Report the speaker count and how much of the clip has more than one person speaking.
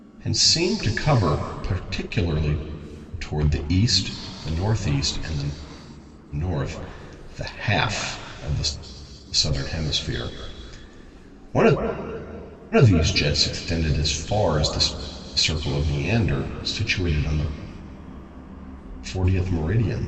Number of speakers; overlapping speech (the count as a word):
one, no overlap